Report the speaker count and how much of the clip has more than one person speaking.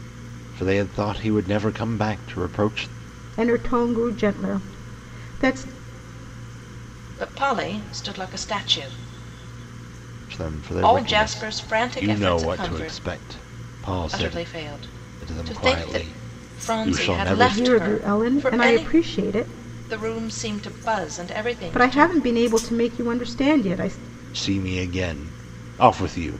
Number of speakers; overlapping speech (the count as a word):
three, about 22%